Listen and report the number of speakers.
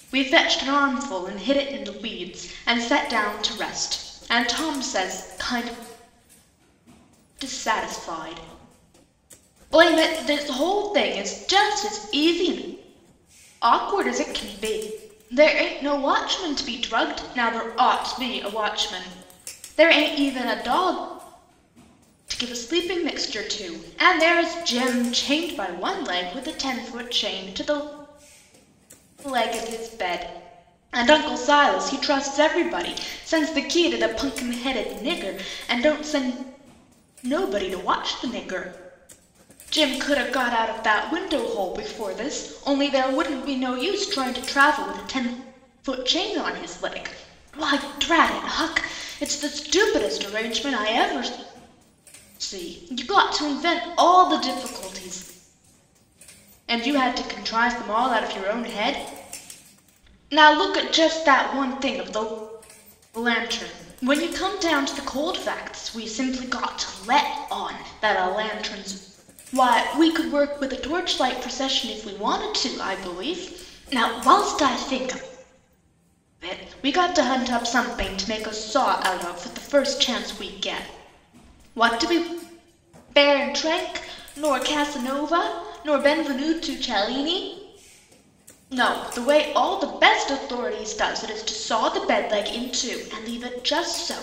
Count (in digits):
1